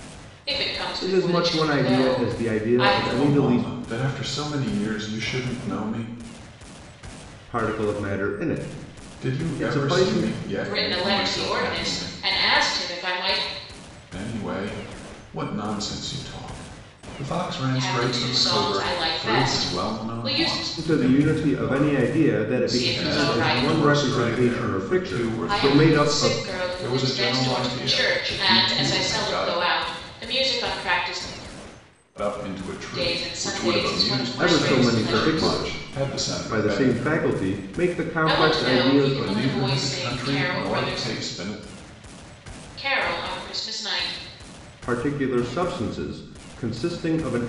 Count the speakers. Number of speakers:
three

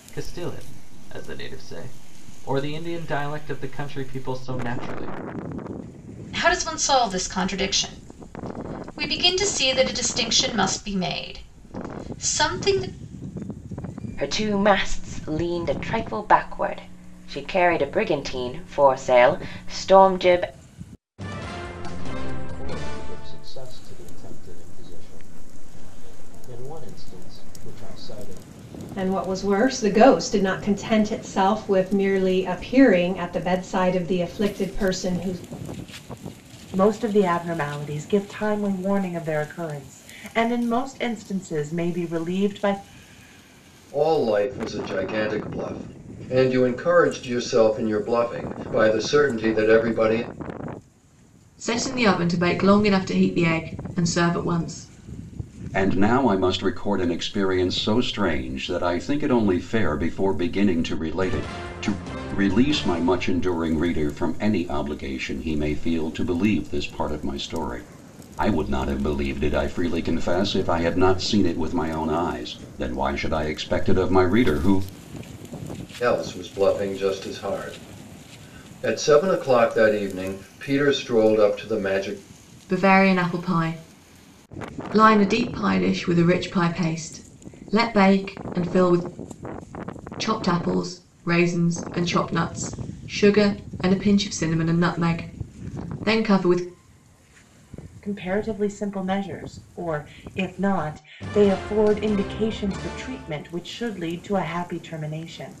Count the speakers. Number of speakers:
nine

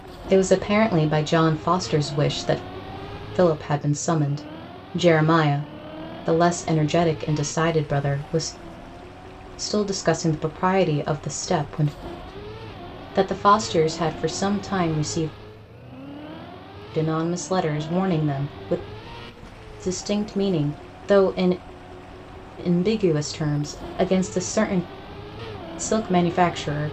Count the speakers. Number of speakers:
one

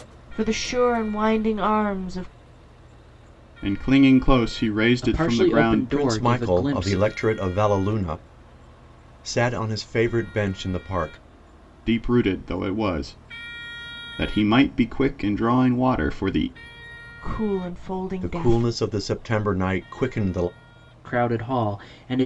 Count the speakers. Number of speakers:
four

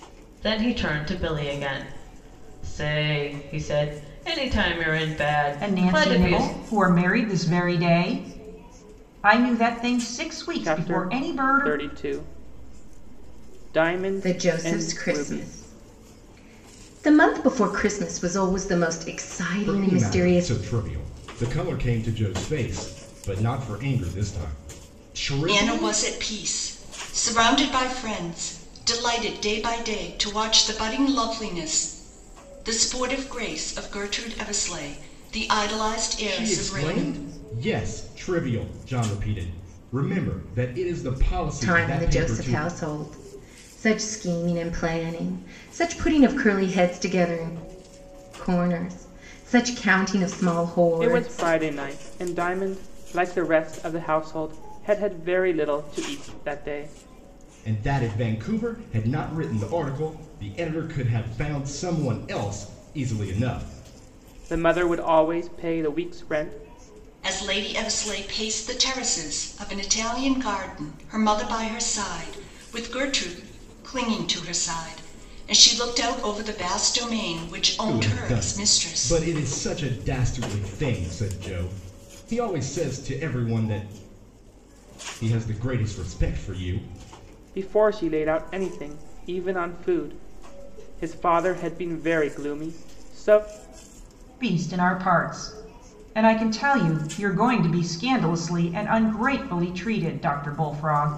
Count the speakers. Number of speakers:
six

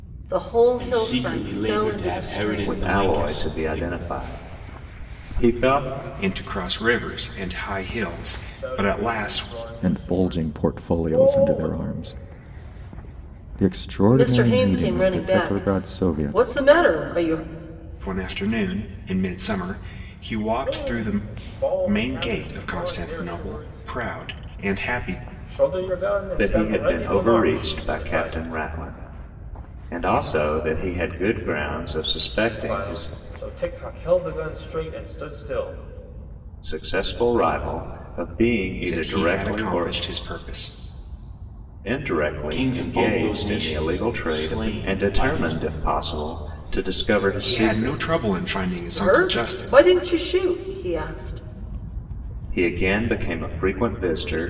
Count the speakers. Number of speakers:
six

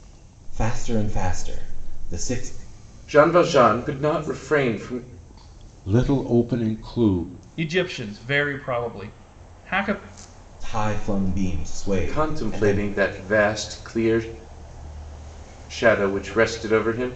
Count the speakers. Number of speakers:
four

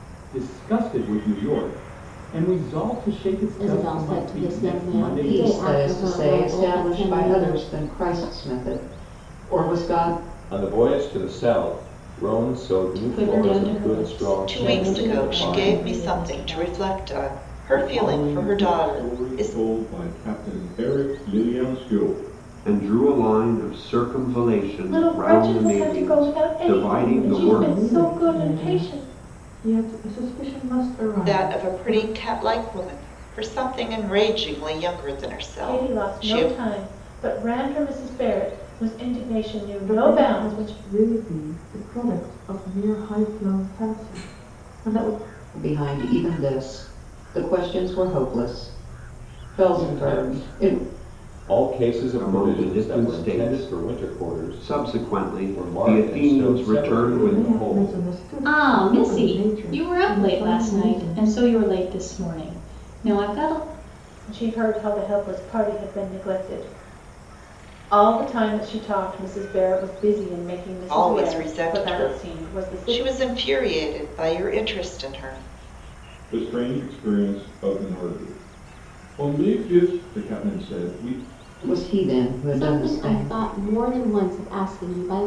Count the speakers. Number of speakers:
ten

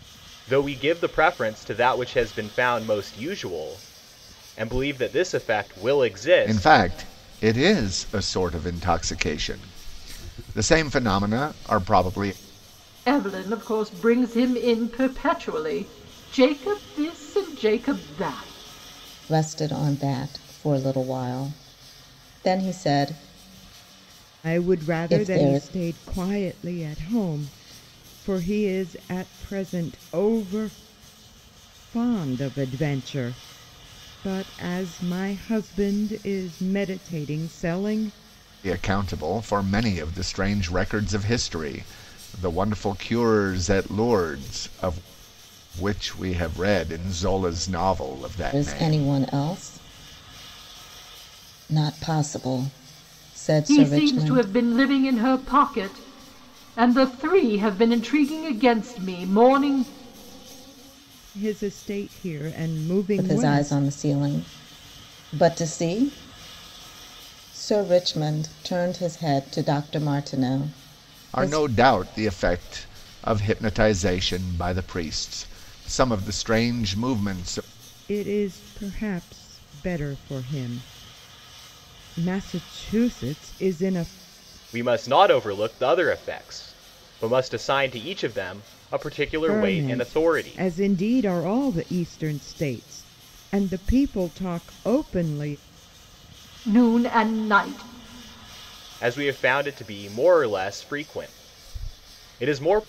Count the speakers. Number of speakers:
five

